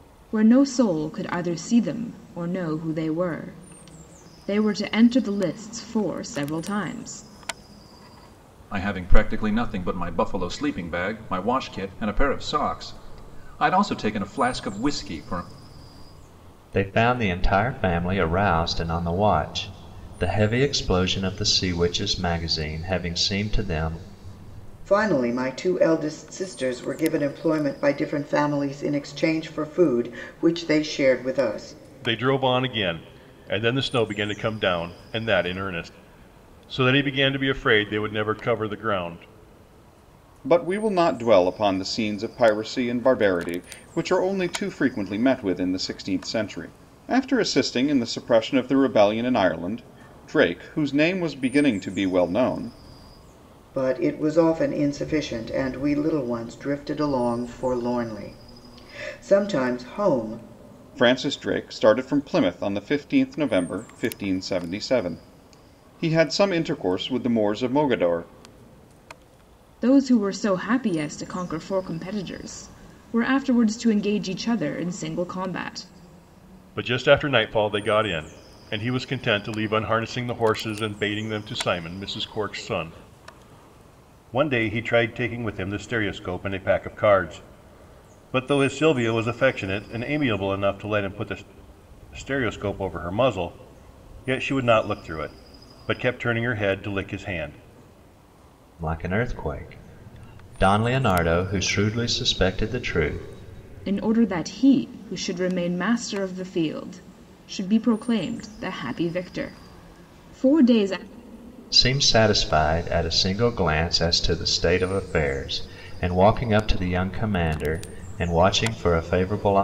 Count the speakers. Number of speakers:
6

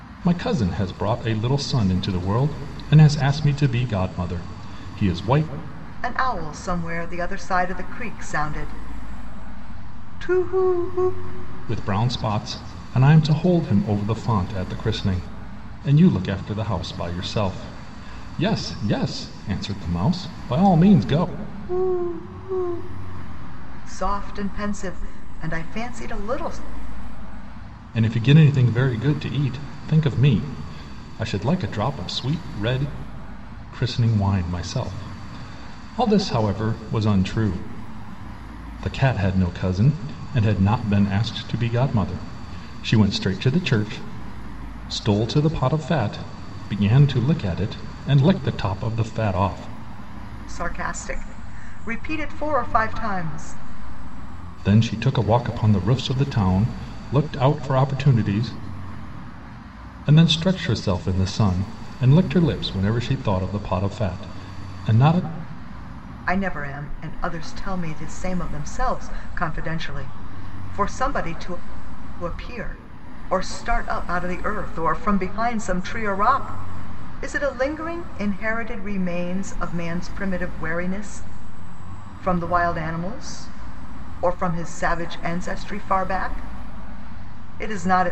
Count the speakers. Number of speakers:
2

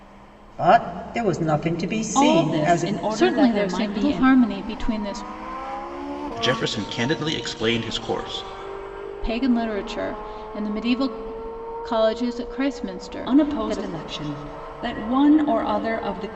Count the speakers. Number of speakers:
4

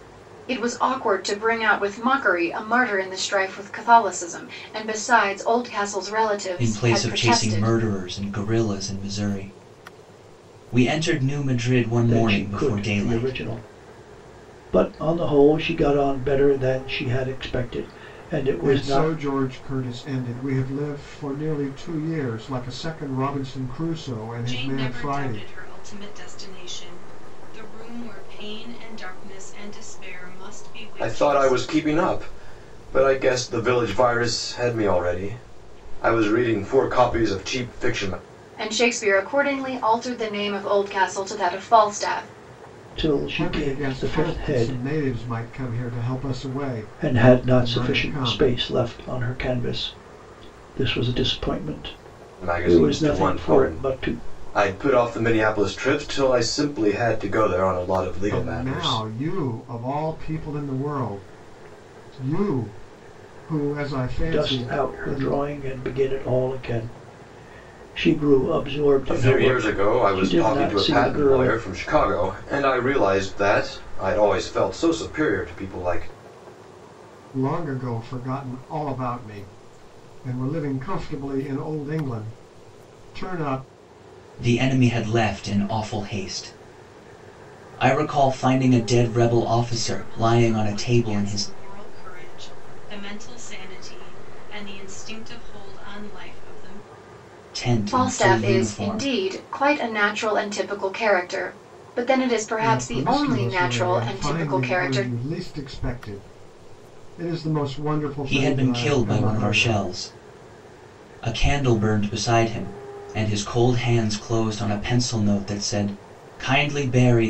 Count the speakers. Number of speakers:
6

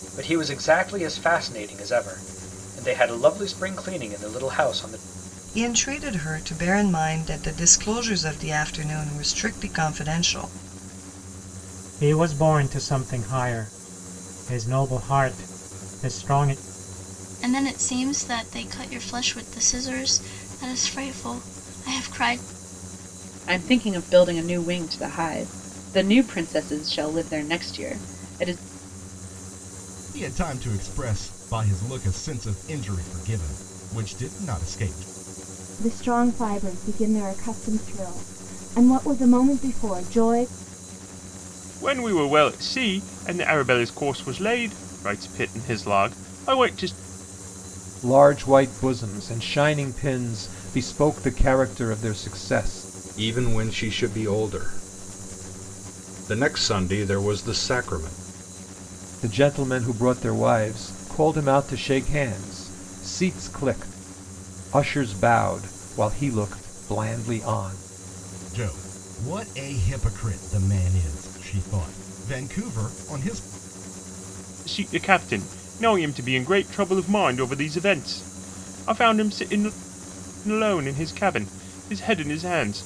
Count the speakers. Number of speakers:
10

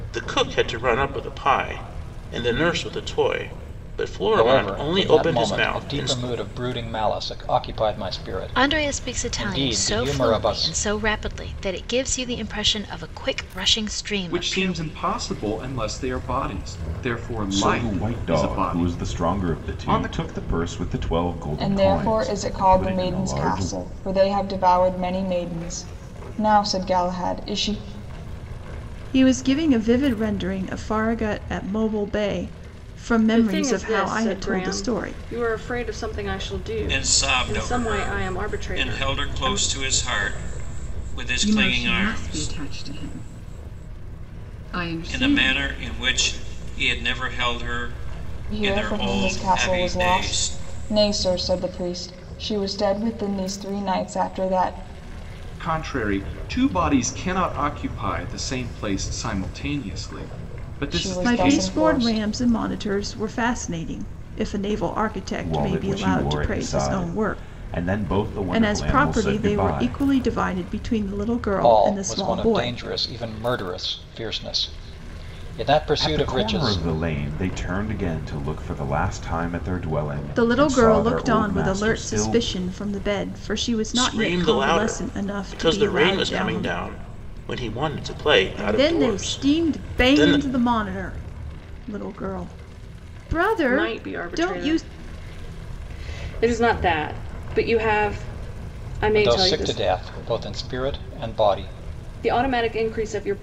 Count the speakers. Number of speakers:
10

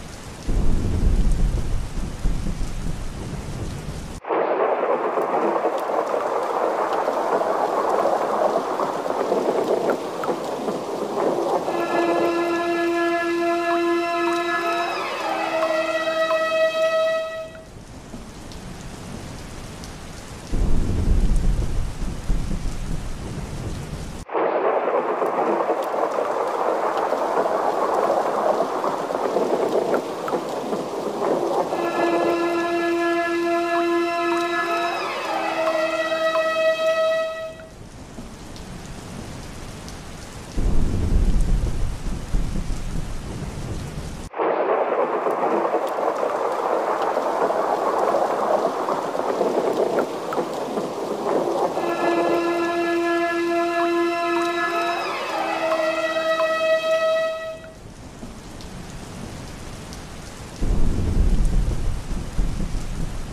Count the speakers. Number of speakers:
0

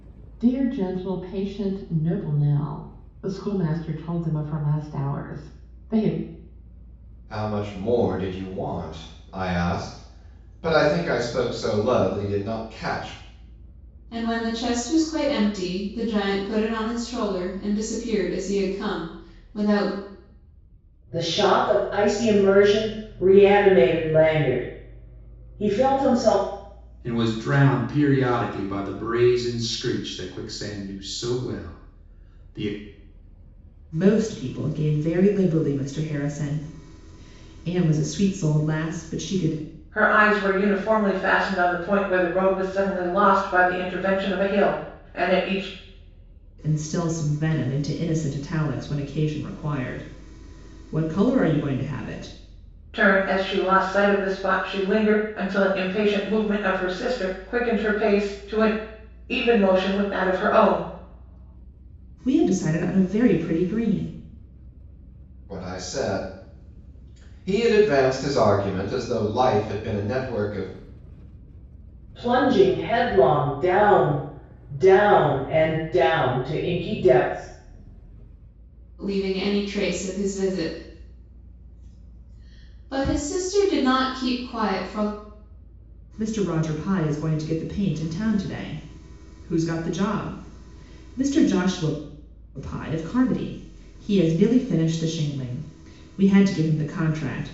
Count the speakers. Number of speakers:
7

